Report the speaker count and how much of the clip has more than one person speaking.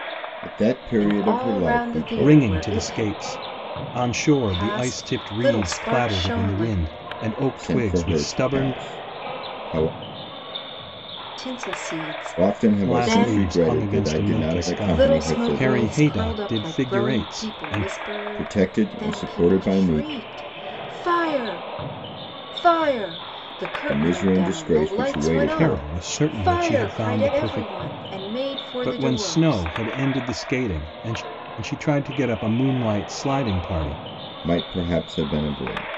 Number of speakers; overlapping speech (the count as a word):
three, about 50%